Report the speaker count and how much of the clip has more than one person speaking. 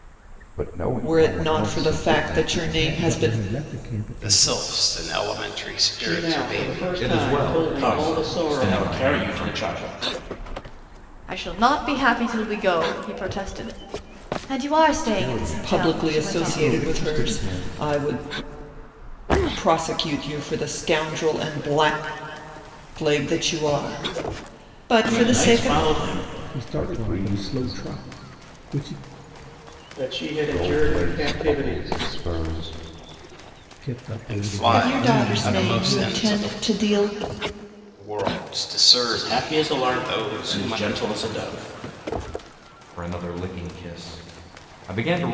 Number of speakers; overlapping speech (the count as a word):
eight, about 39%